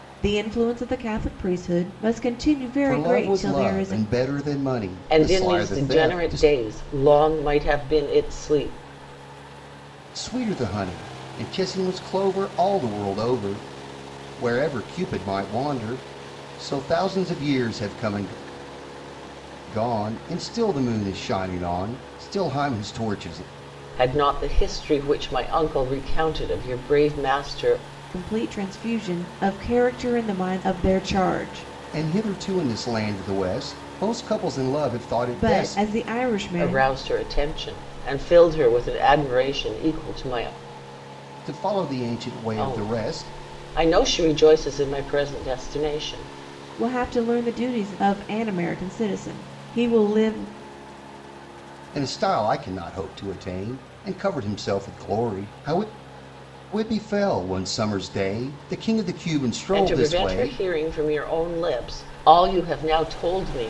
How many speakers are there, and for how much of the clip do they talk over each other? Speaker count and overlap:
three, about 8%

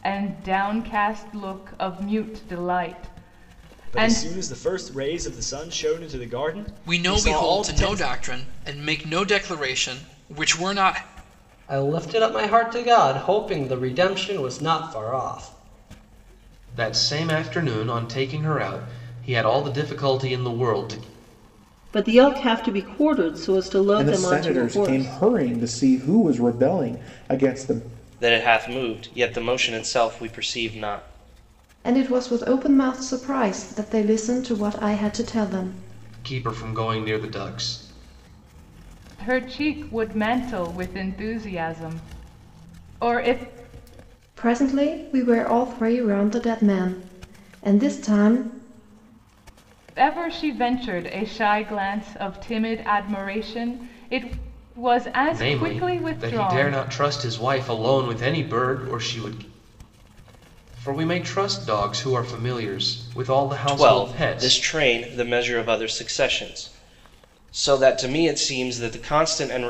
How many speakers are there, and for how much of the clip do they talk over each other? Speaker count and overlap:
nine, about 8%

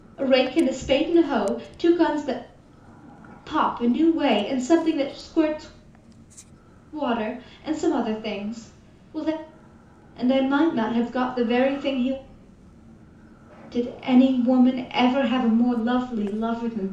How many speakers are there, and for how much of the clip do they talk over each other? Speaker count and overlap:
one, no overlap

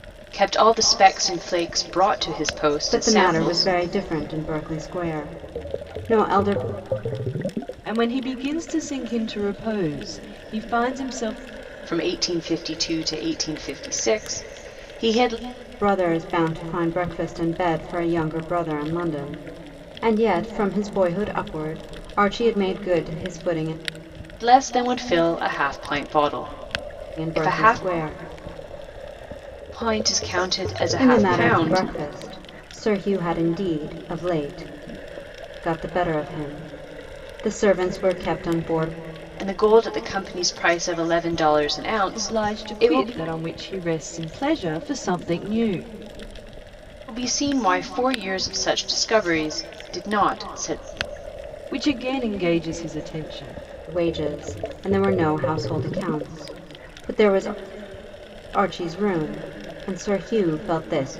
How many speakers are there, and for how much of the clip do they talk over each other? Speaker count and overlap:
three, about 6%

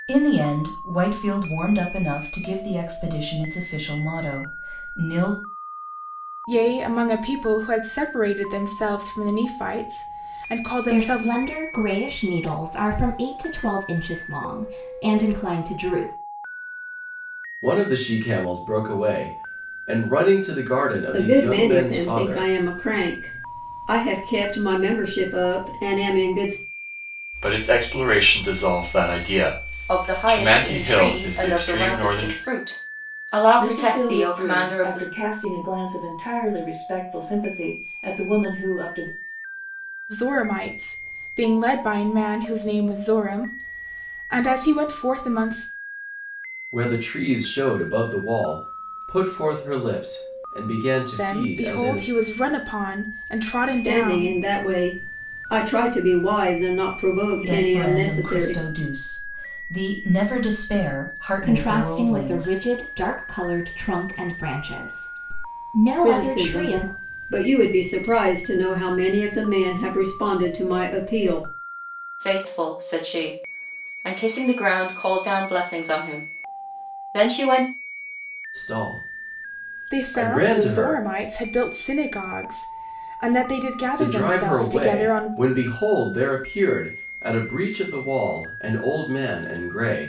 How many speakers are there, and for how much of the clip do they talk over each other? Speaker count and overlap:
eight, about 15%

